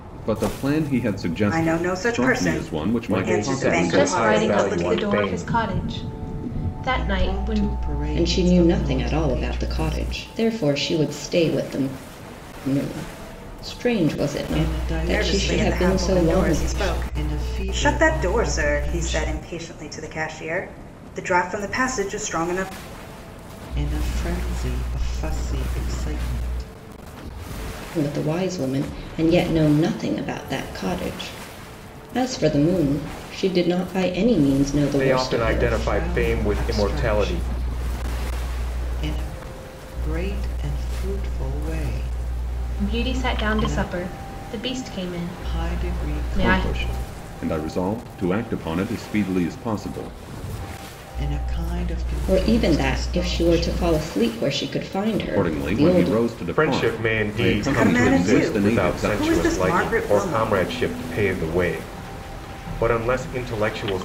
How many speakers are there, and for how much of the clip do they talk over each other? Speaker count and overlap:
6, about 38%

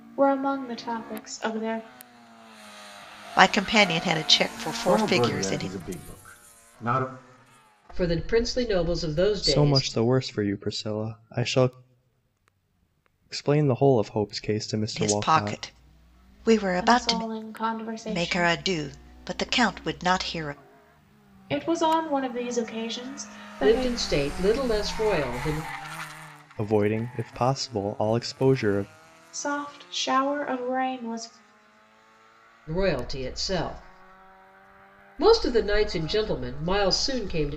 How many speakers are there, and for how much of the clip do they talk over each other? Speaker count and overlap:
5, about 9%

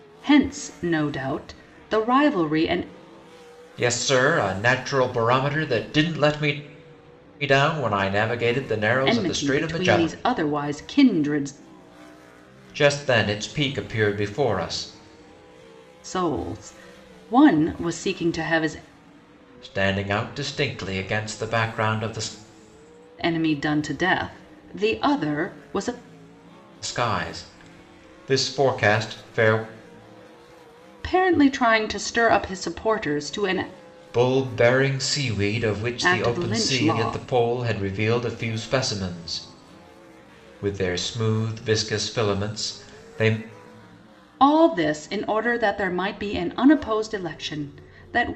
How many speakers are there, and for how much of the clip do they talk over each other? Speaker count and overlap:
2, about 5%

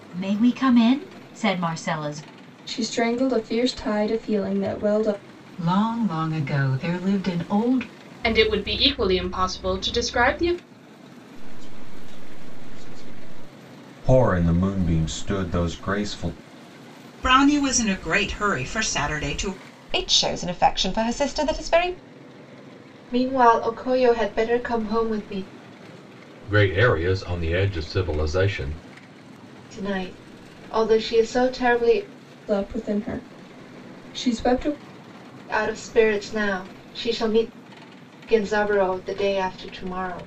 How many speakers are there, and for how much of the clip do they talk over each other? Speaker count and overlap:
10, no overlap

